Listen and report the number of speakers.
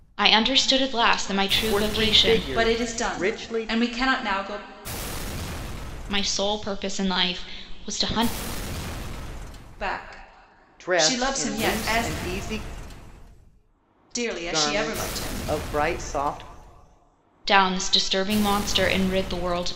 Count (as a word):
three